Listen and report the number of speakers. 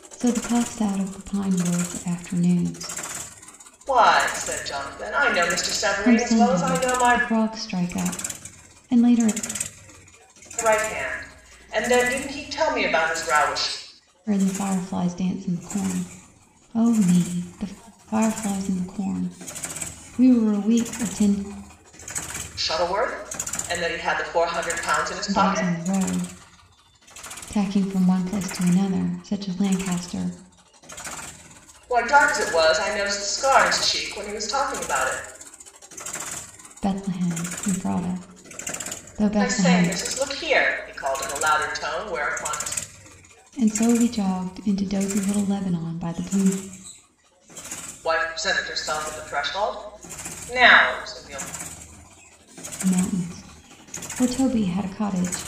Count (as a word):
two